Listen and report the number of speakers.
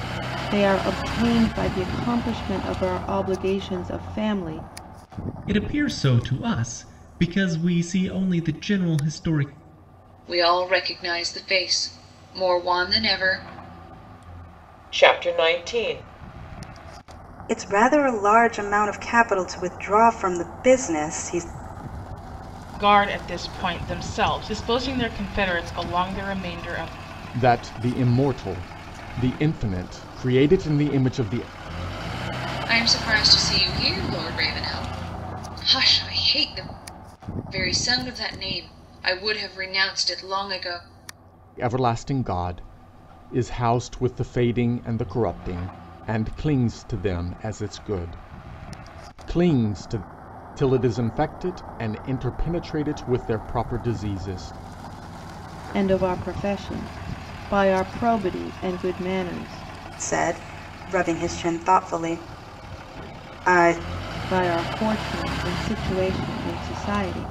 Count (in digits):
7